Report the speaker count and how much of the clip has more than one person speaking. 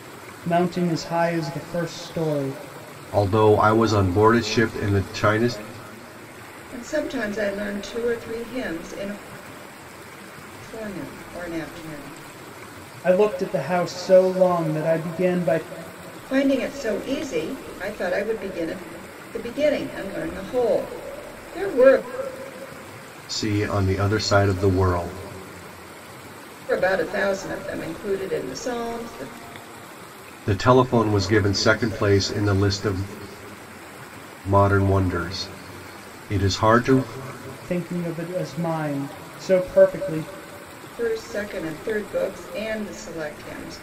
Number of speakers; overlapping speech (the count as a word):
three, no overlap